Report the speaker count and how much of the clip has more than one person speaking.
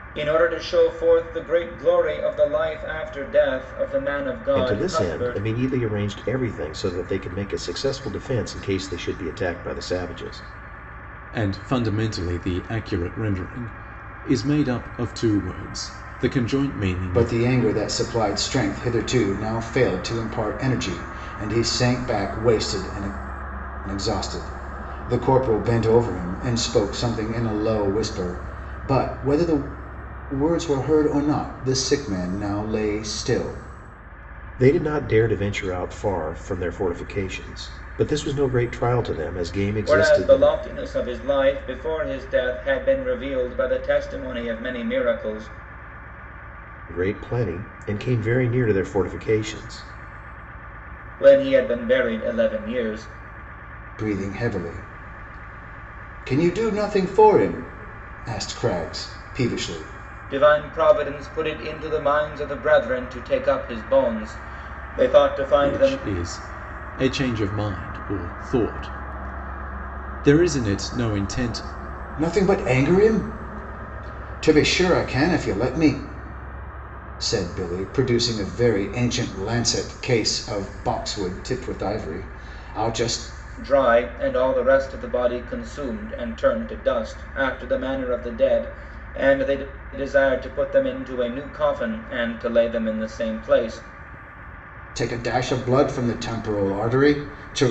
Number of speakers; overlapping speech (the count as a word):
four, about 3%